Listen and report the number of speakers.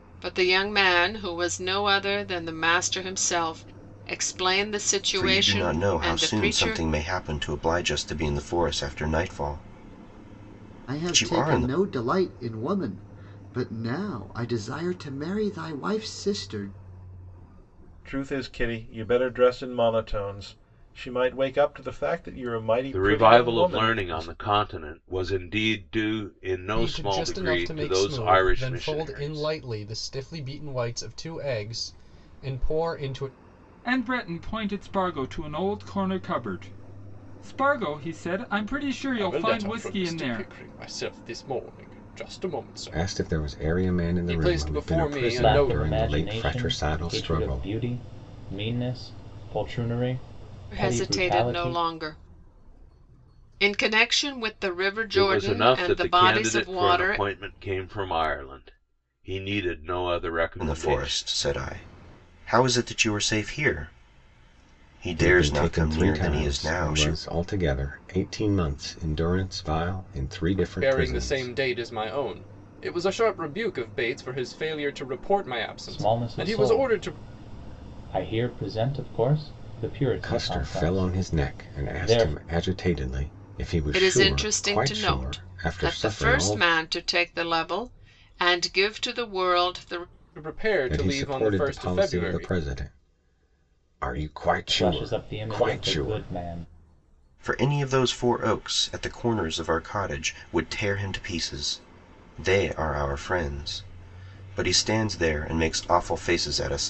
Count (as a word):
ten